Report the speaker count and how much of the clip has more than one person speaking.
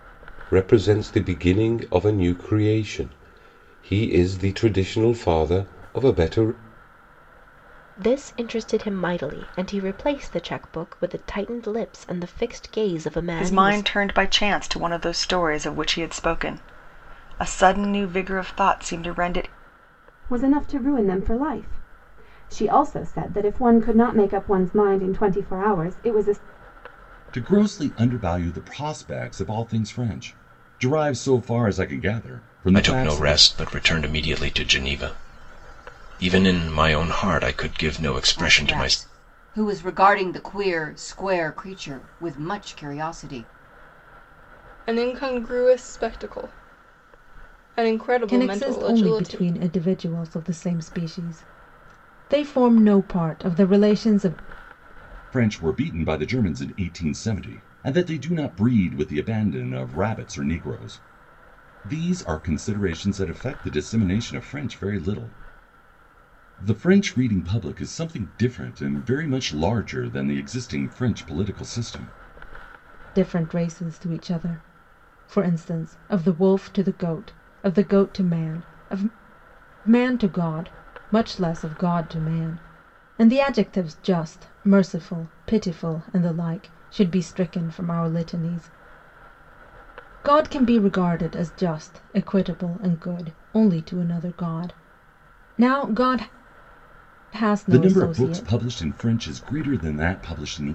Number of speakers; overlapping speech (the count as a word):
nine, about 4%